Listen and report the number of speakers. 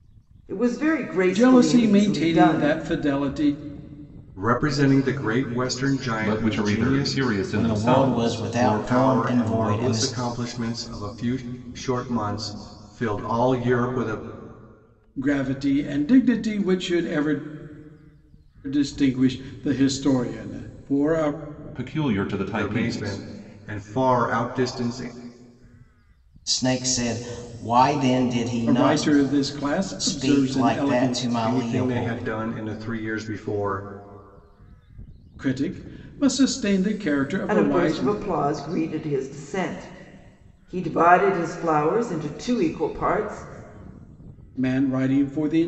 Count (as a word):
five